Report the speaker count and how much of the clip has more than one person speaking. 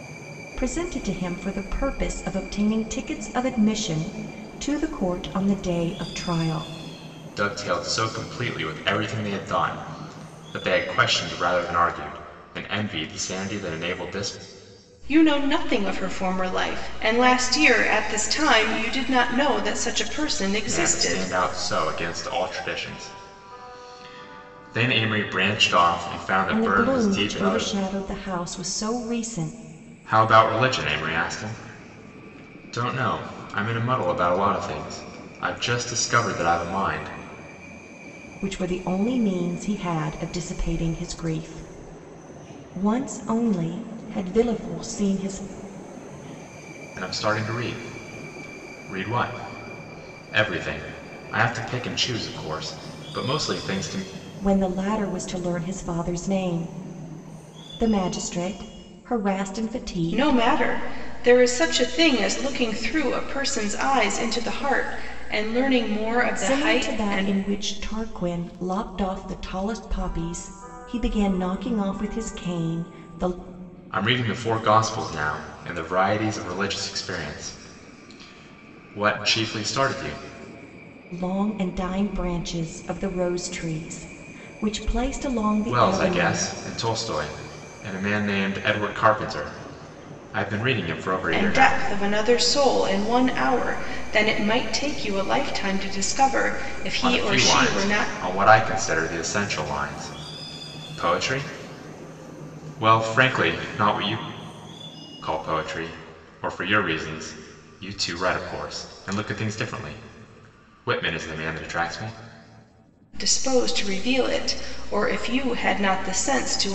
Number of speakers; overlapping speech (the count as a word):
three, about 5%